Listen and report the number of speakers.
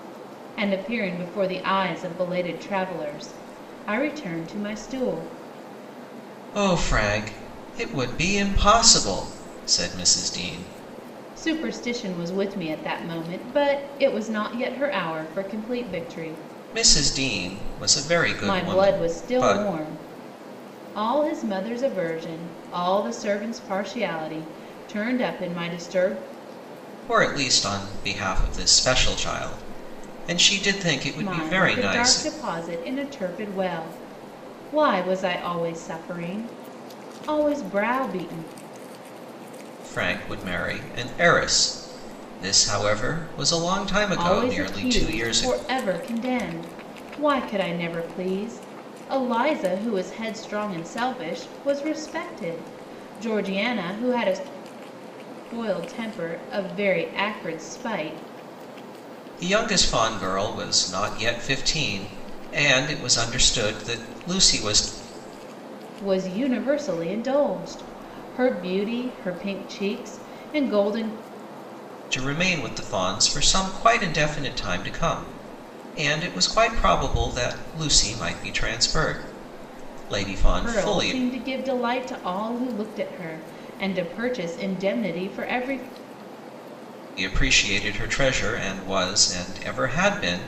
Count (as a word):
two